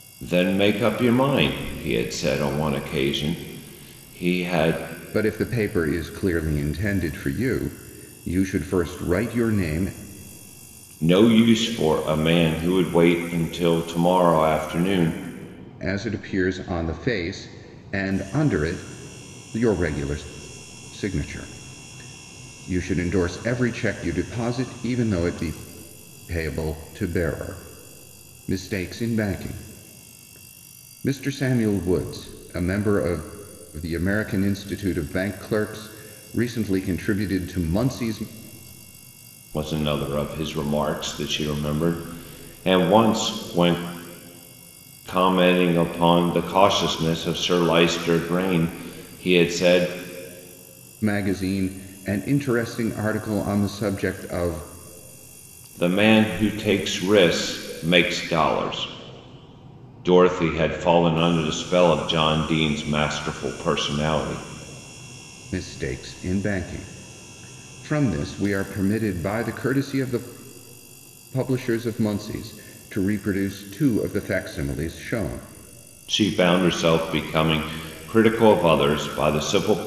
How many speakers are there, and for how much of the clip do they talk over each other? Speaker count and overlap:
2, no overlap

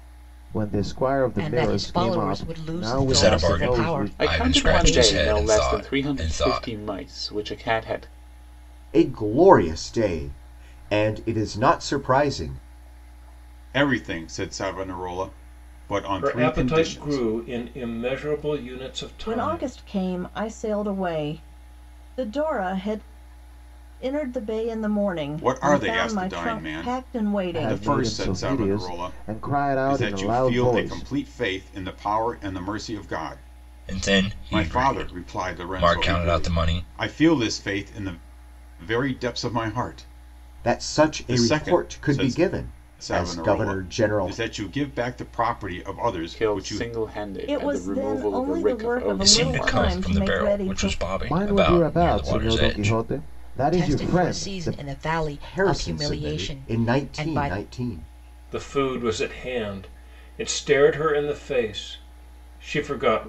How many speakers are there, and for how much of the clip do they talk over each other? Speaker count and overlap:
8, about 43%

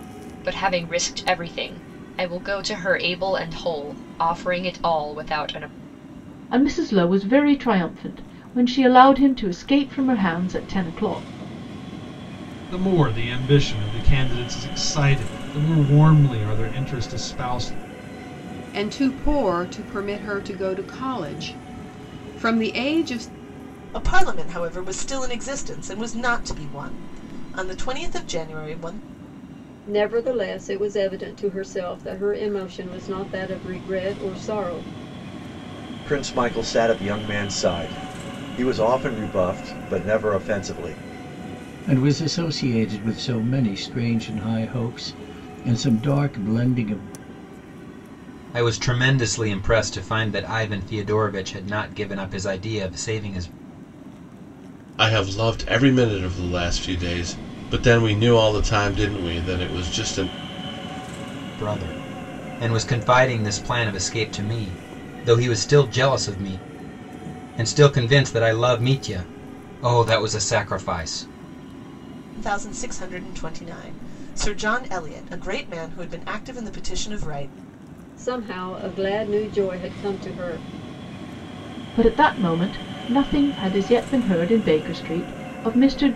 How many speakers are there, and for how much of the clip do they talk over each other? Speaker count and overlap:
10, no overlap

